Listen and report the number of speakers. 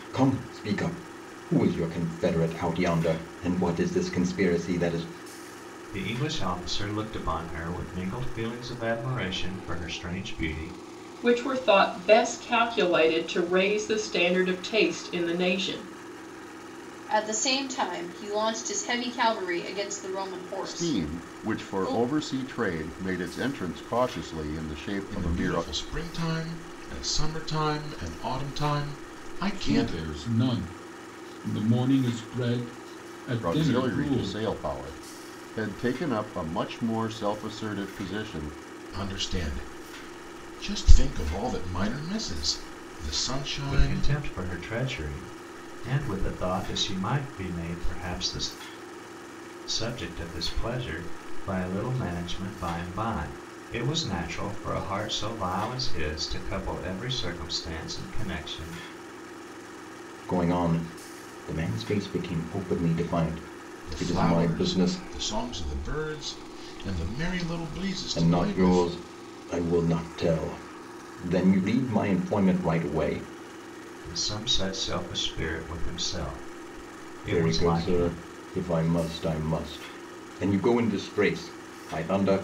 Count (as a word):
seven